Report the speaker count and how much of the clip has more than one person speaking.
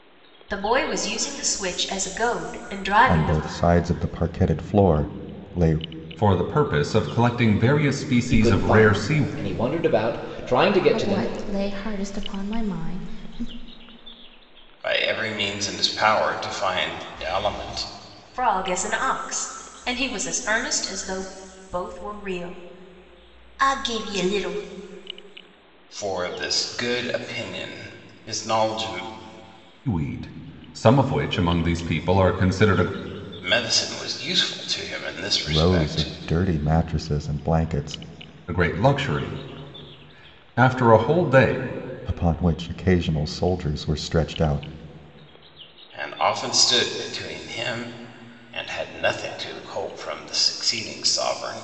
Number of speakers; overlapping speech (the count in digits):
6, about 5%